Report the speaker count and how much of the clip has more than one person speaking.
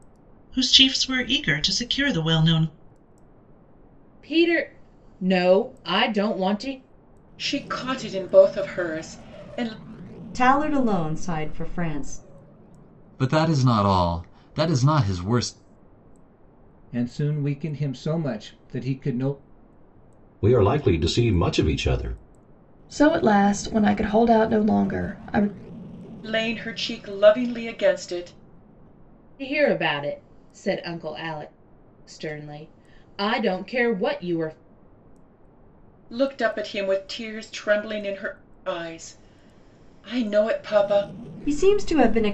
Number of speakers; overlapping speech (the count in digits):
8, no overlap